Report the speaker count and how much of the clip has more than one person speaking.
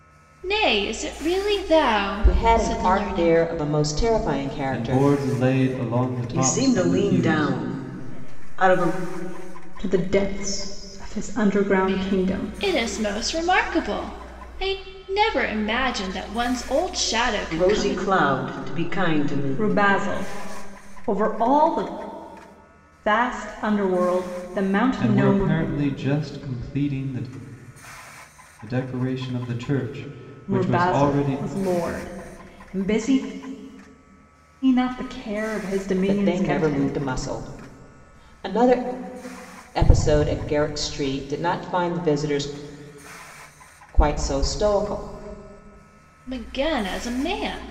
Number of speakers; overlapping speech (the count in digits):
6, about 22%